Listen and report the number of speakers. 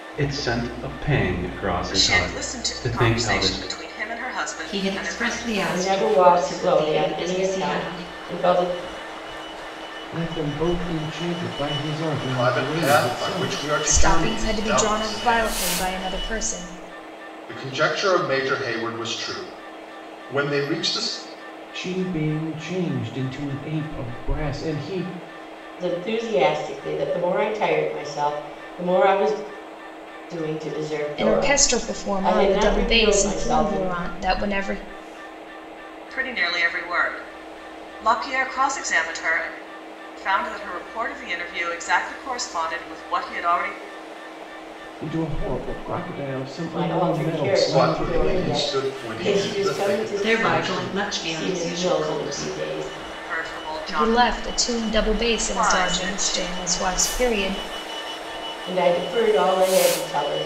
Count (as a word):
seven